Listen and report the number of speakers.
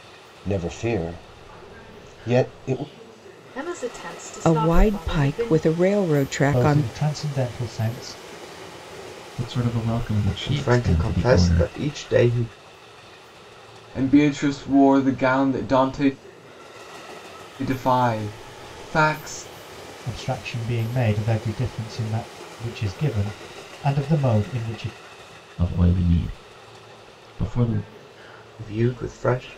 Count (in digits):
7